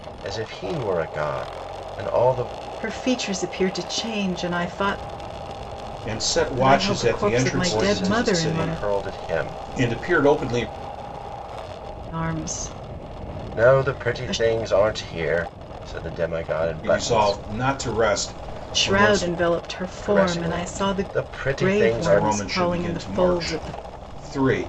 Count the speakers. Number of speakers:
3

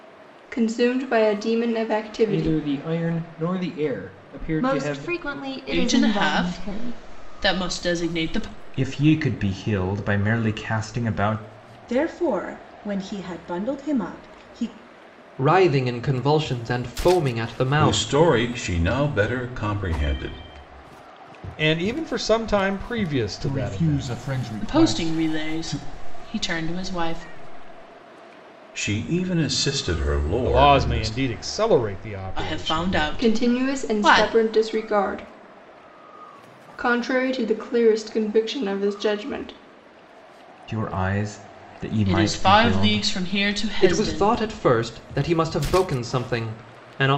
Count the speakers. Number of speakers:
10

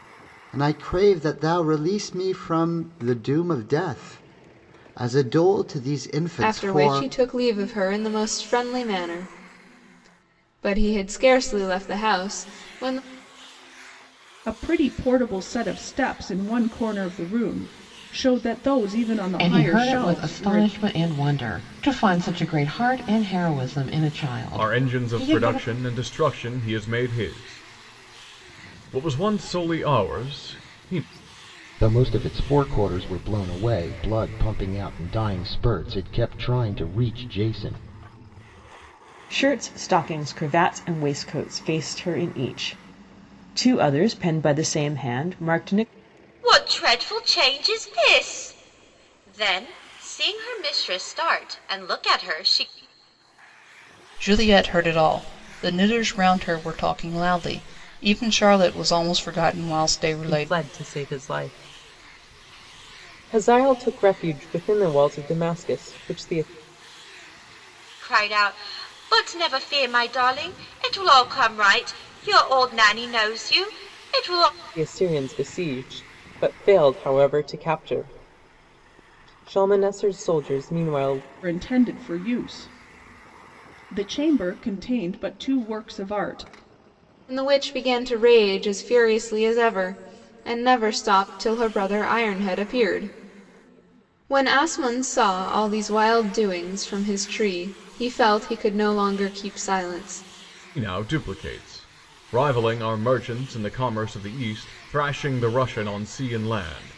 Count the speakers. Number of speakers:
10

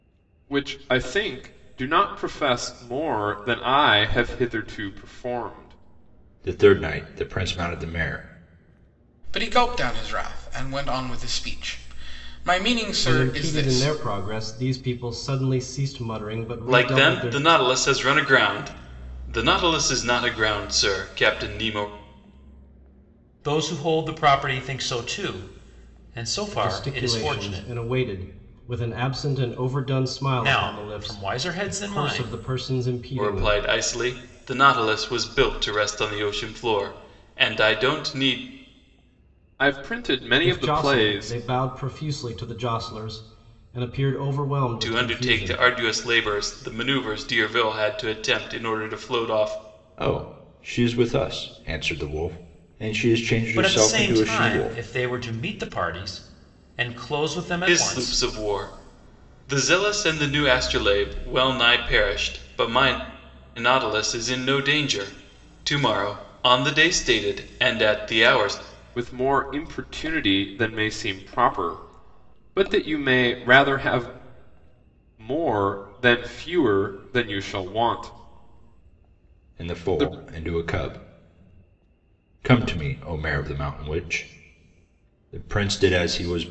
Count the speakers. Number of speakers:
6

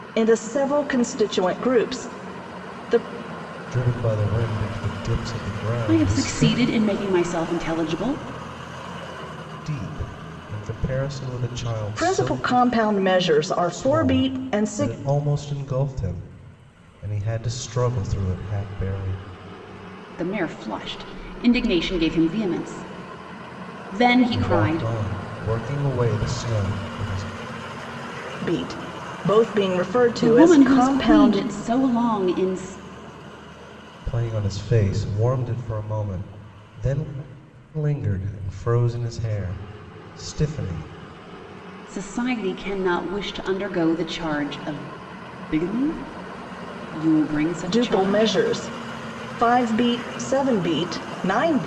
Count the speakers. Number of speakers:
3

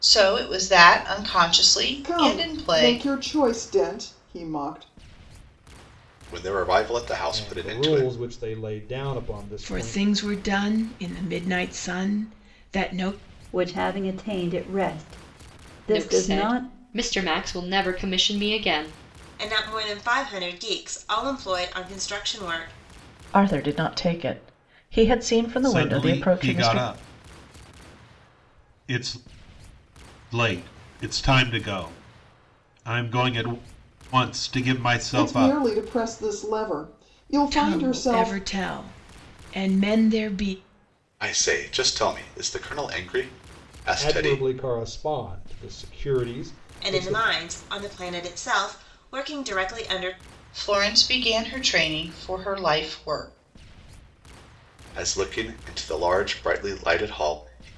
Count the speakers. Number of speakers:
10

